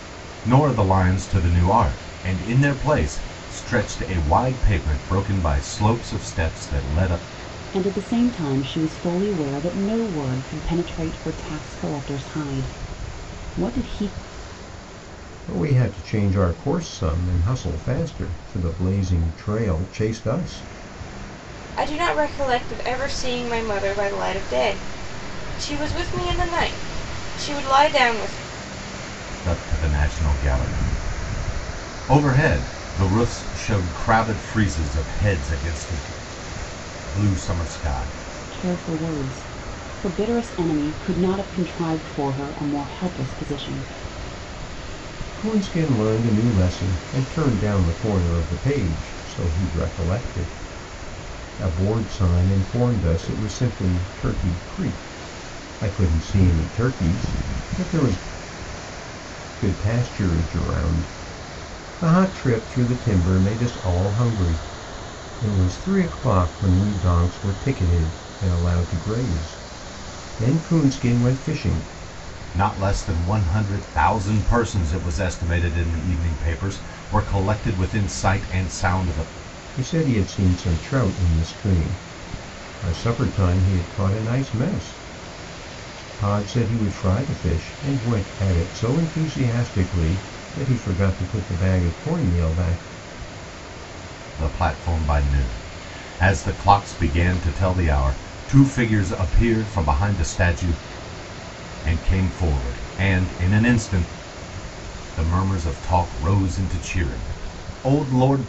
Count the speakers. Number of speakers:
4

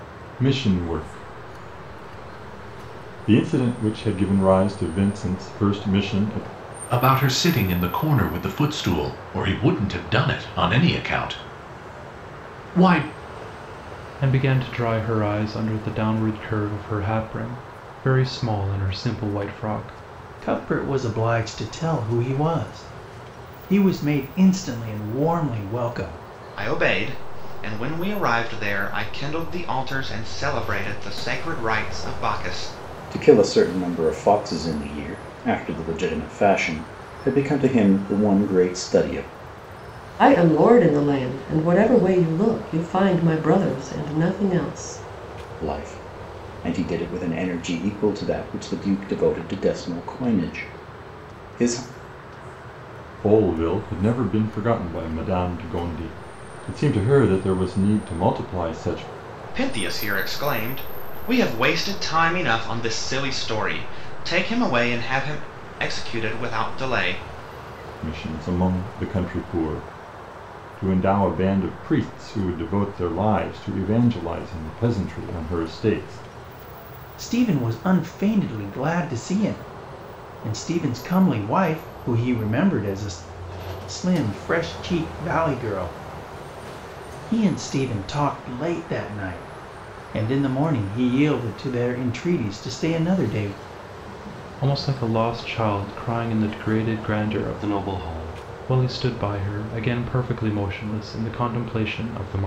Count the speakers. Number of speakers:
7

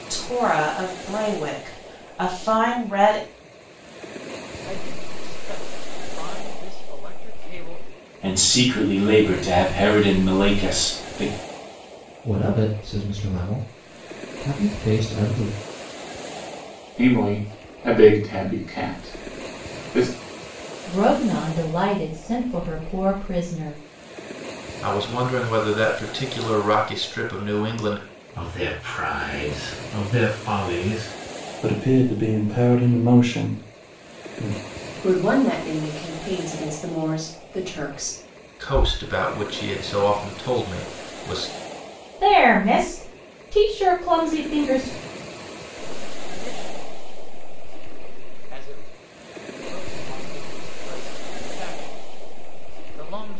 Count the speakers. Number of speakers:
10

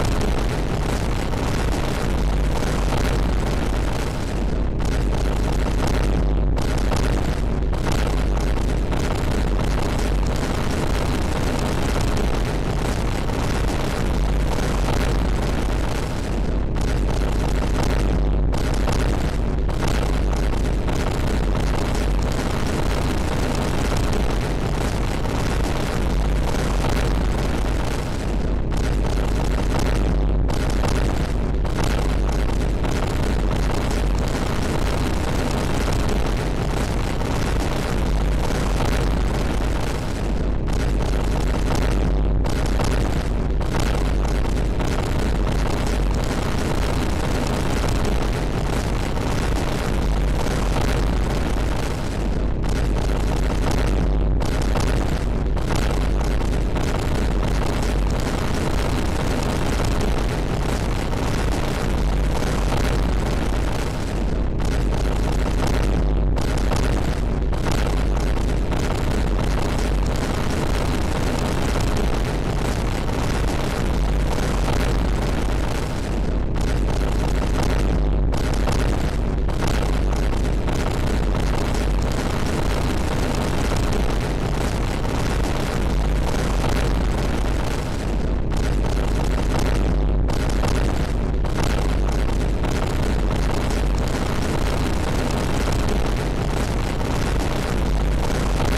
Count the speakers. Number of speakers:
0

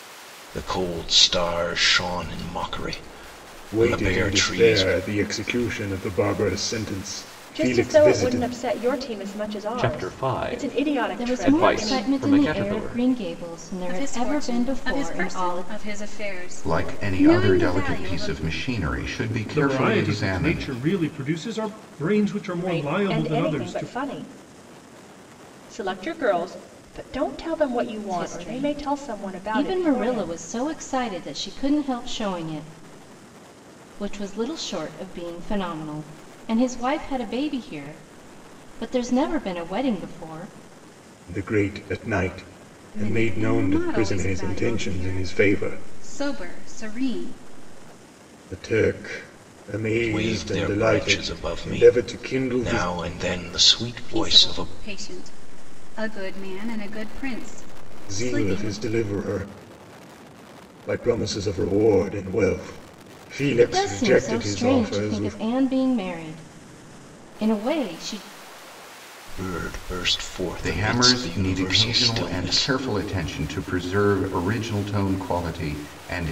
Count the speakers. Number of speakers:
8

